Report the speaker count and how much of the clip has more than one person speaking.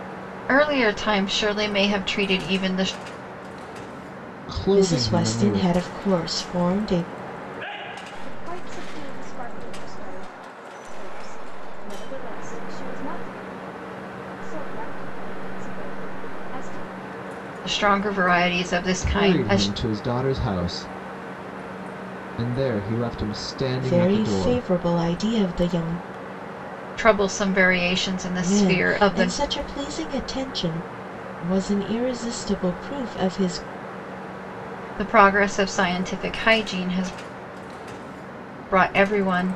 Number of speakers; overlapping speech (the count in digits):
4, about 9%